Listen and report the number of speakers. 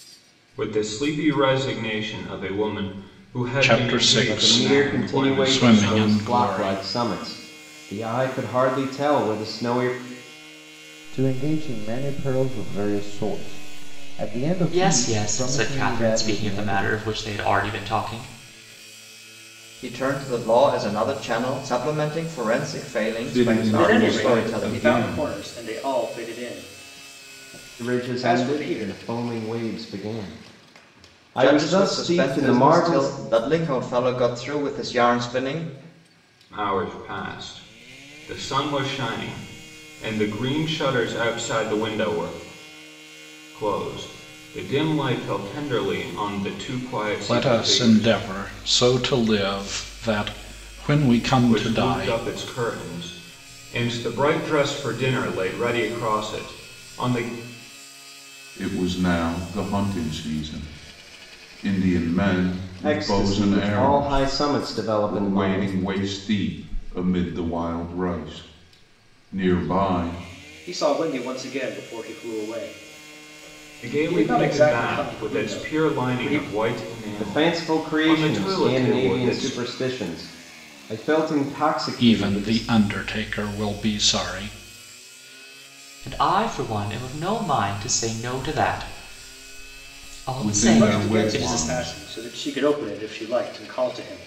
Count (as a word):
eight